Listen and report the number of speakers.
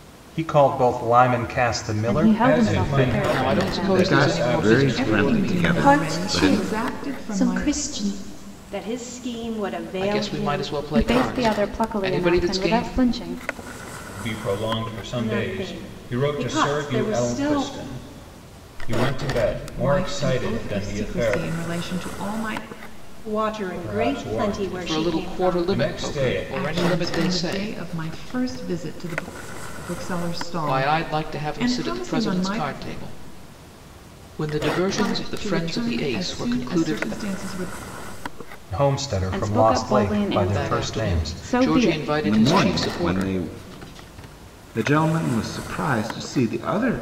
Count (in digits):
8